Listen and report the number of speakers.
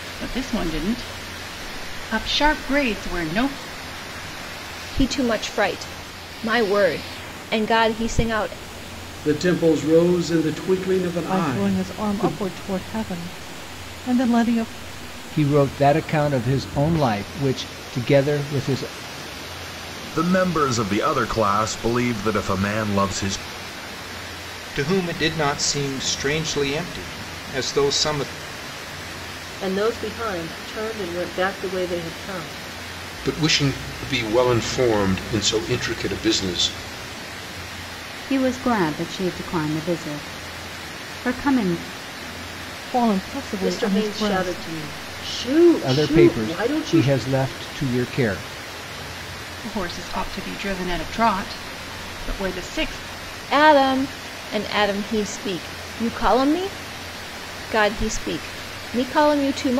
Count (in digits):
10